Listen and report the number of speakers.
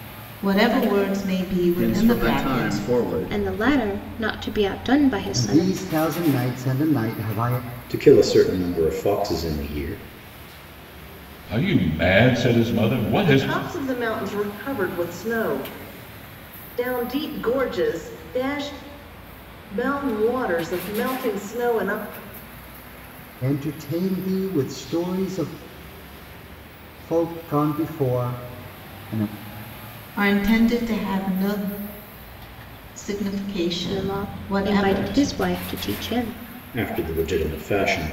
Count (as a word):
seven